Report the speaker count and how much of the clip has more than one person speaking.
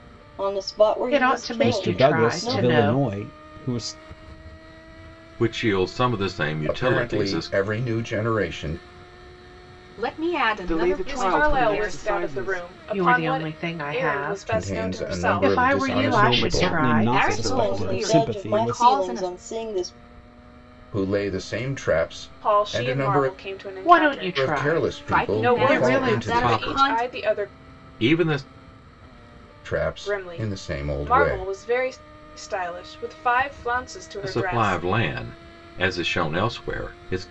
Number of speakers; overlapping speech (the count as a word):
eight, about 48%